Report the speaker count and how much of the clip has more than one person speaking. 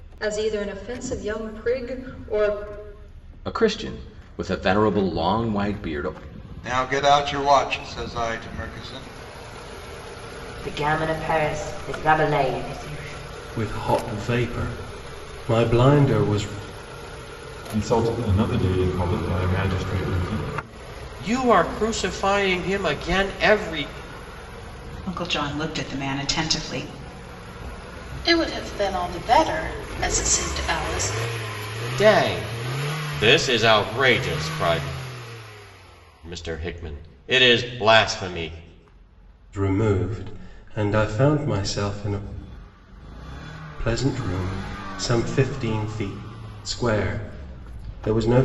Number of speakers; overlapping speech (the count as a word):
nine, no overlap